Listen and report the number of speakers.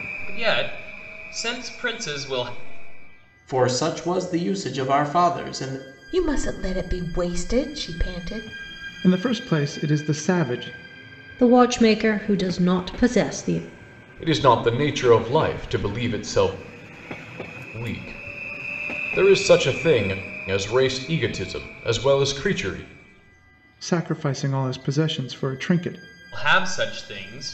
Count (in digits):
6